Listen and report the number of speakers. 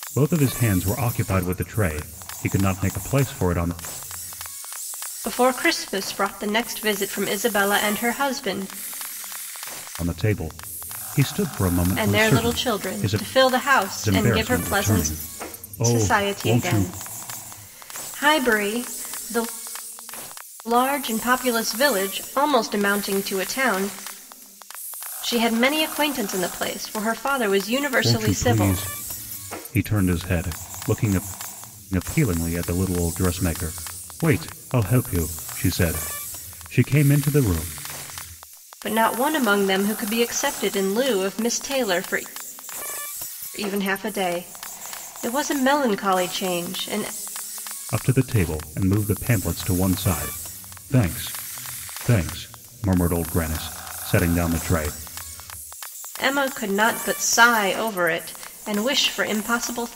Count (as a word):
two